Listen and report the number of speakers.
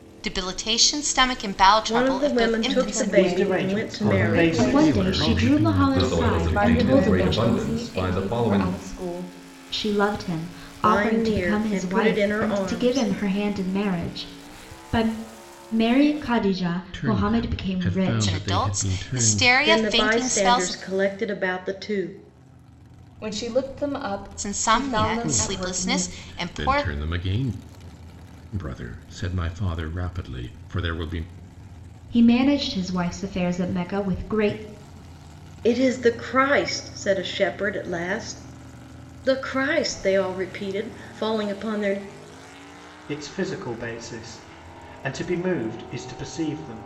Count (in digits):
7